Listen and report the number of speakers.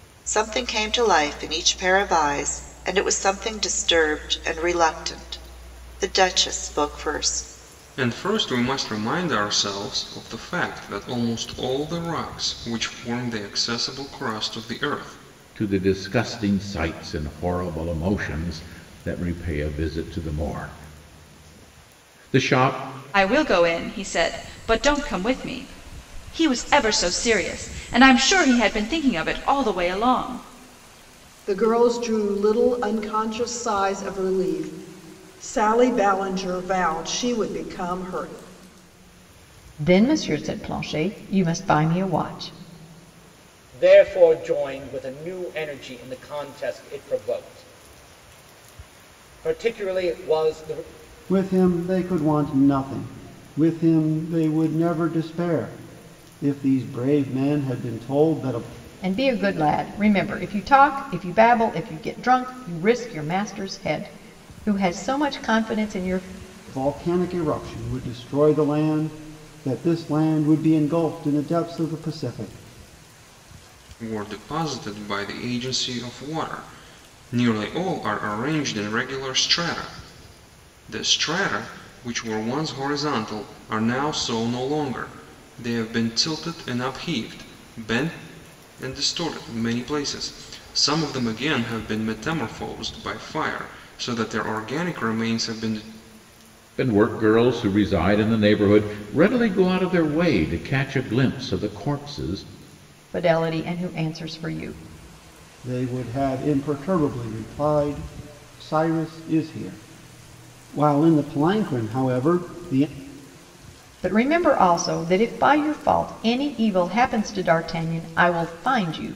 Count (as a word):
eight